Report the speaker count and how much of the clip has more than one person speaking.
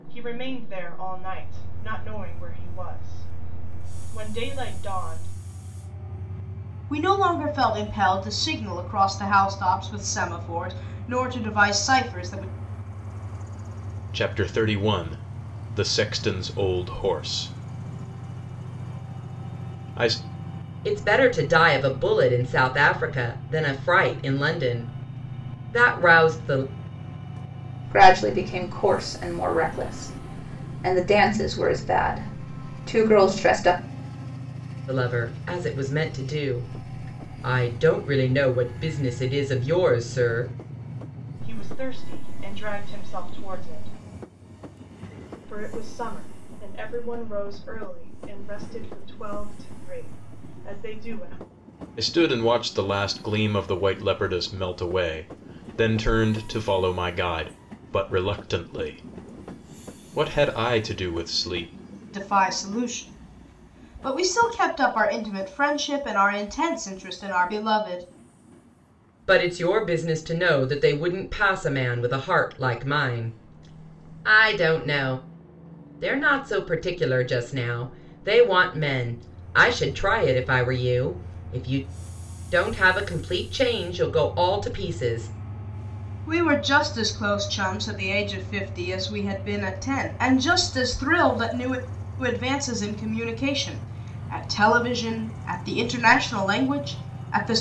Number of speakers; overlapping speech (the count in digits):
5, no overlap